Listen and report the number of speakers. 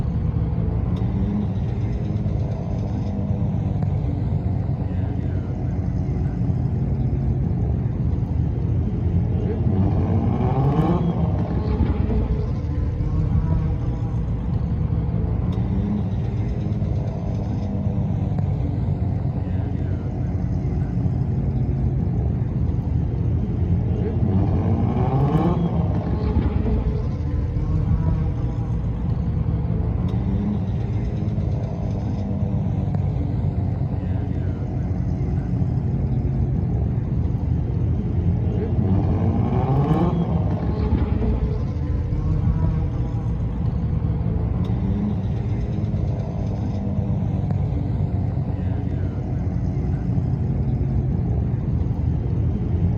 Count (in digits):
0